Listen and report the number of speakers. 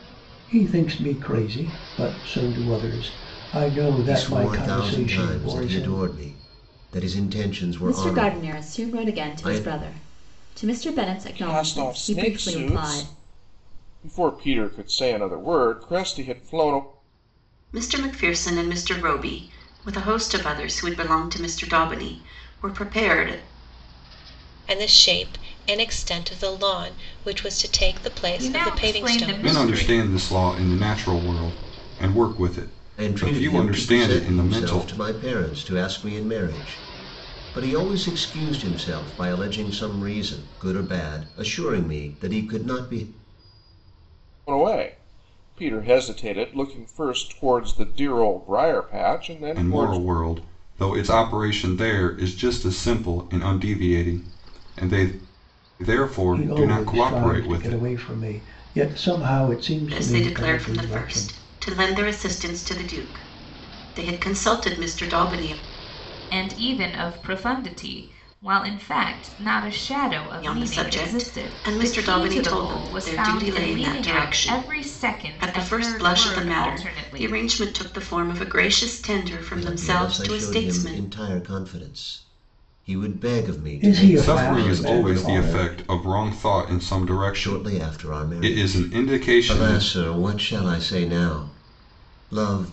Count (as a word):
eight